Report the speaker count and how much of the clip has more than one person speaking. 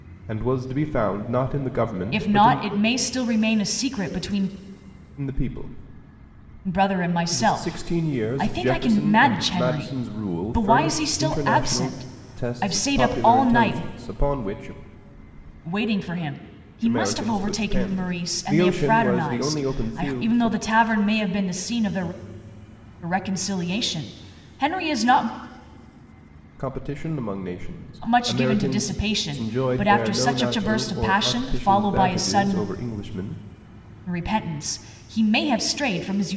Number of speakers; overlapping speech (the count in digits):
2, about 42%